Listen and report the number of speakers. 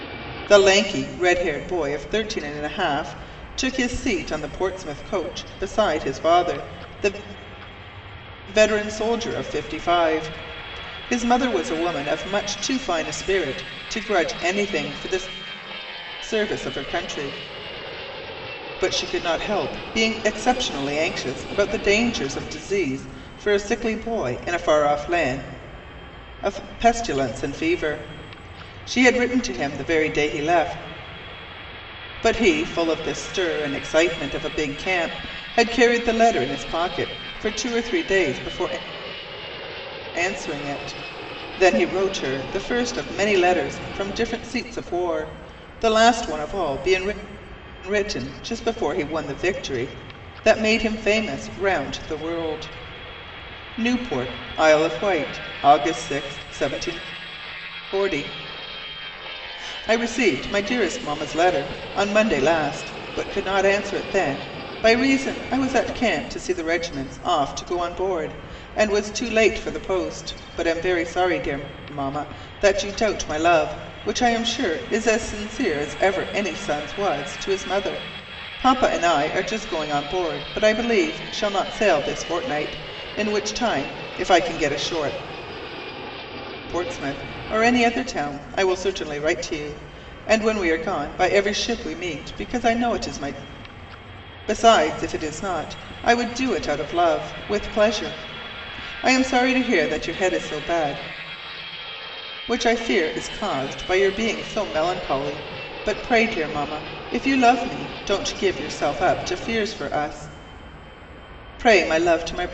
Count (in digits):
1